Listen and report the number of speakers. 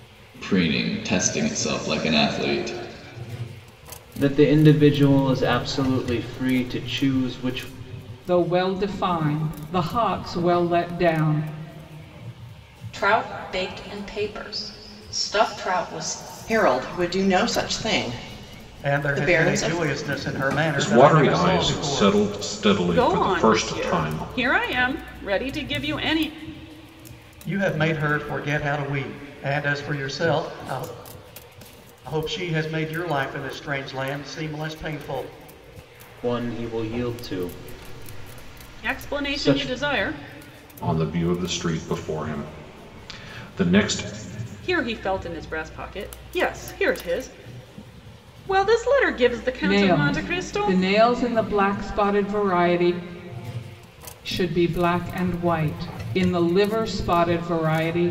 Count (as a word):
eight